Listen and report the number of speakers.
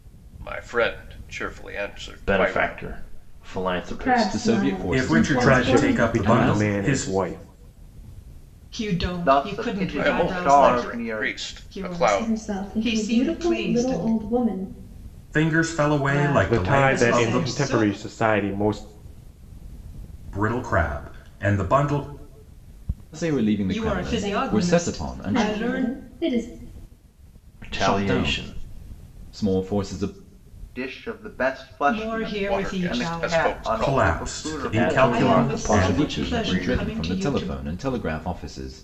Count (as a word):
eight